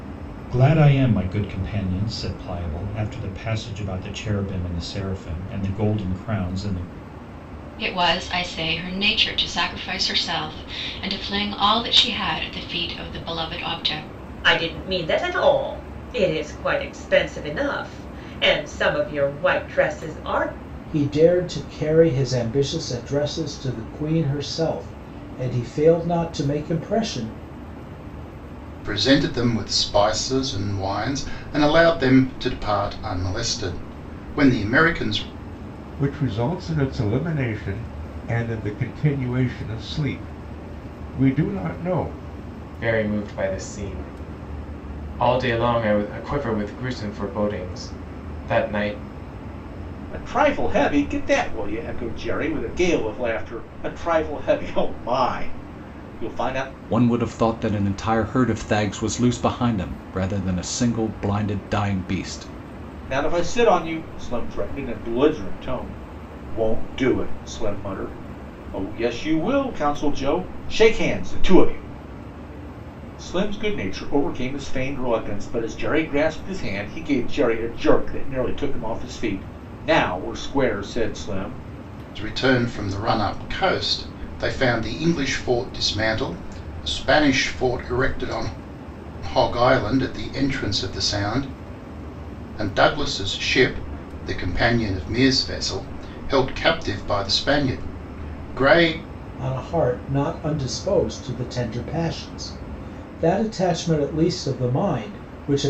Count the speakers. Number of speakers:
9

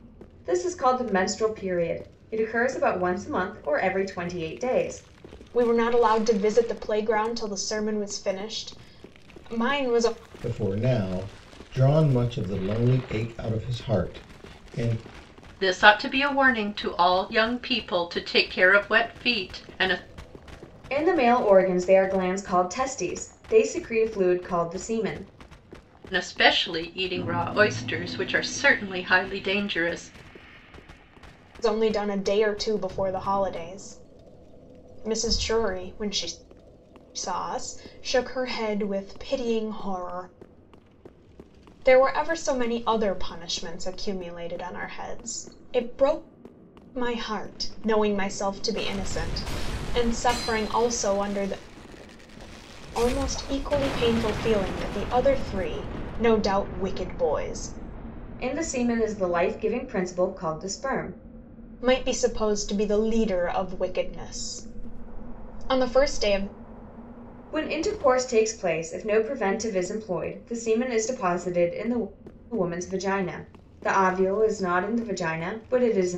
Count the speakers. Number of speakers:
4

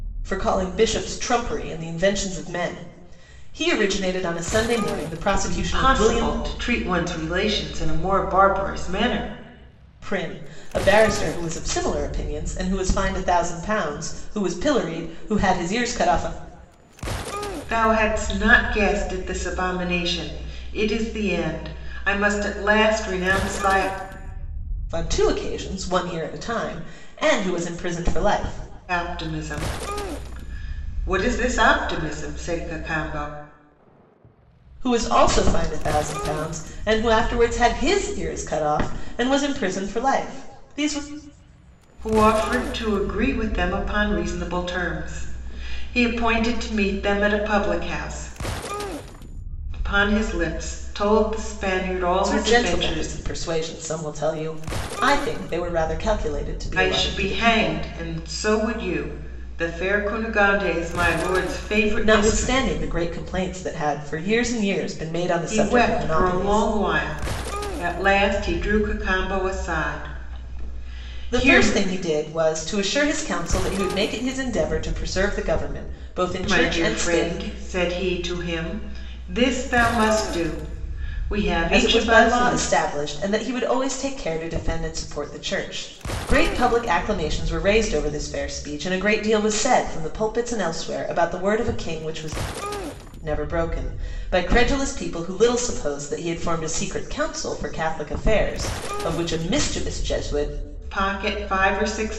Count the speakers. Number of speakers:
2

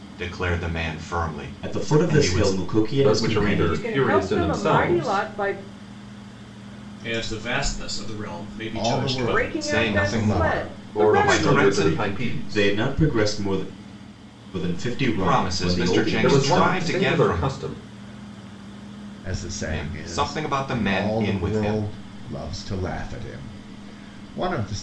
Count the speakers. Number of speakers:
6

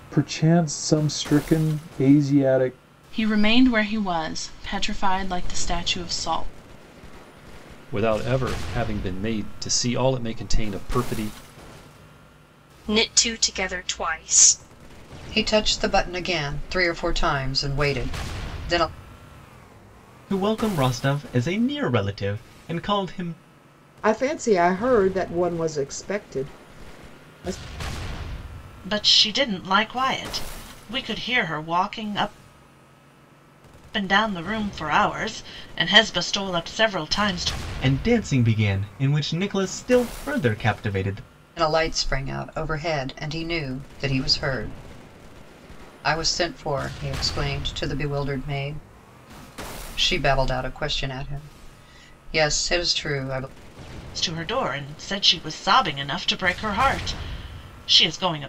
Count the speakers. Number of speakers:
8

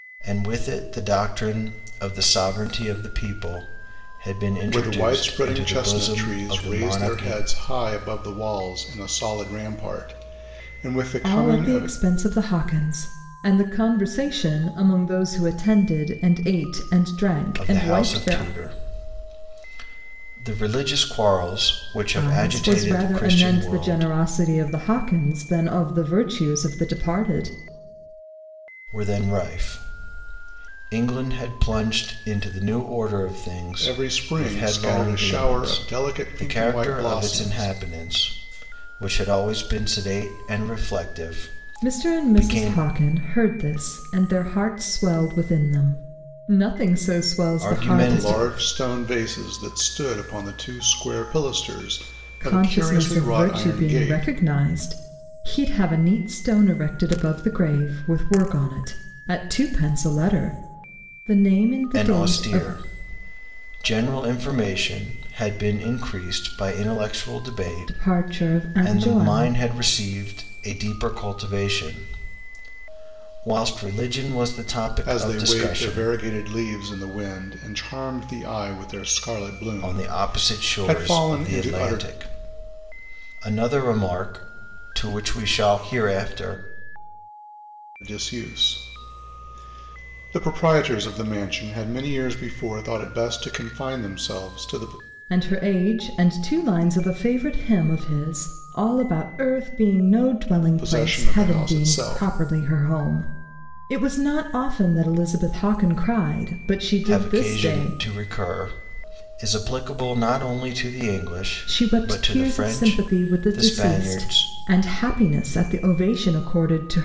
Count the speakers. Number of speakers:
3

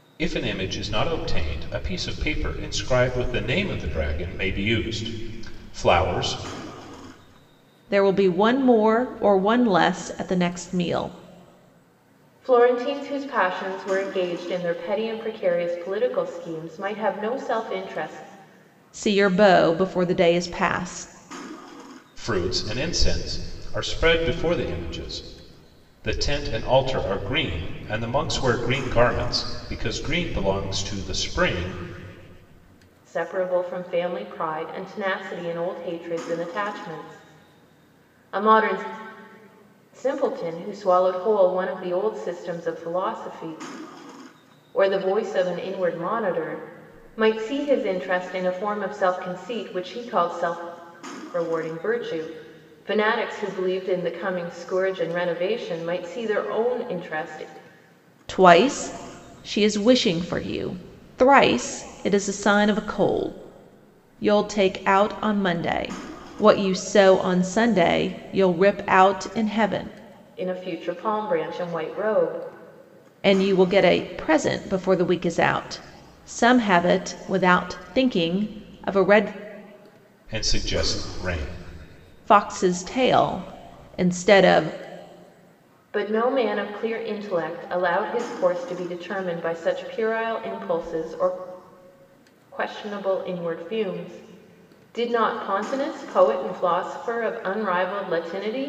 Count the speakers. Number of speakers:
3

